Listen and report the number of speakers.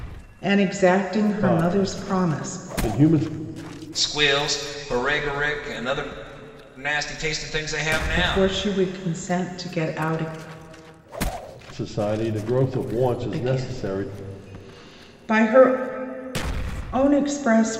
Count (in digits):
3